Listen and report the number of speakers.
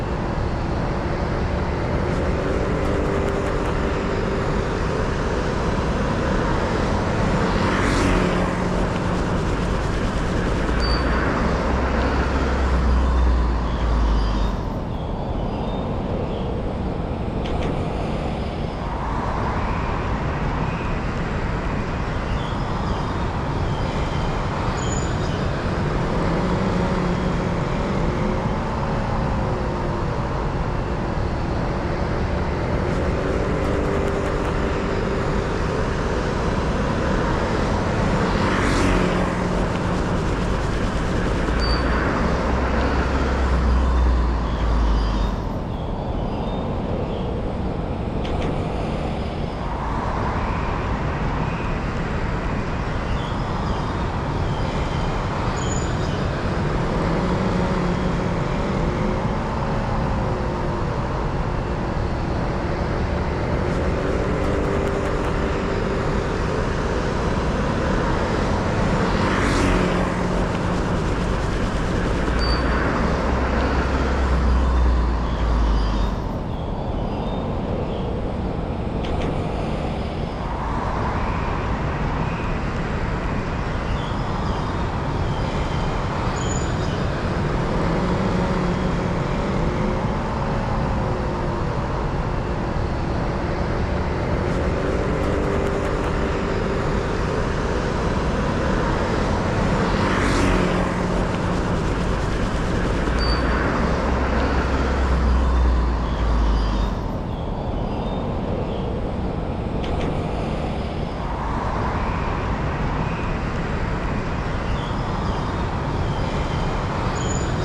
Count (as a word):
zero